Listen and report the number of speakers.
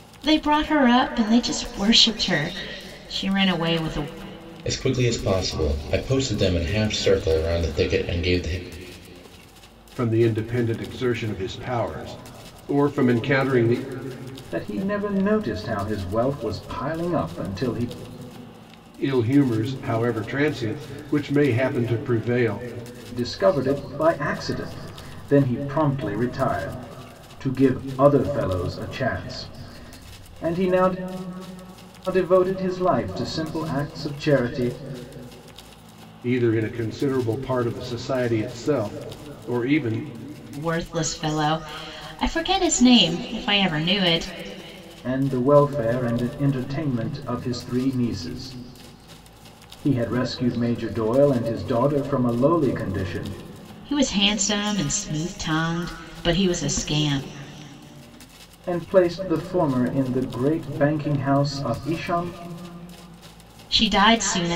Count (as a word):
four